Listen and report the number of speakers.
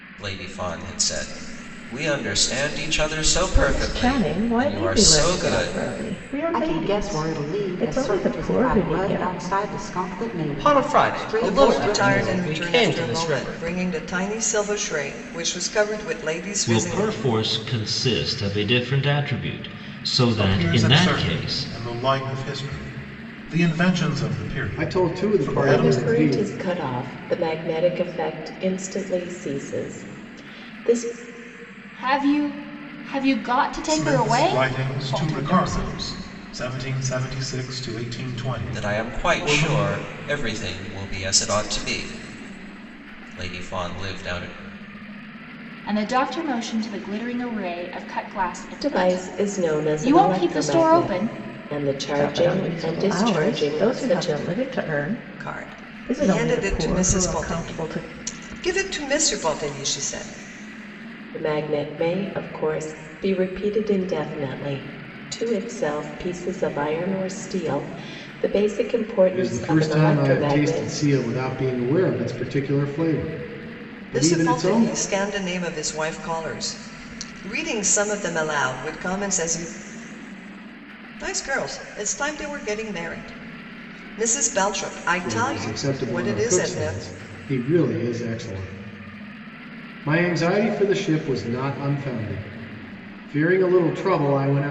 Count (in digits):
10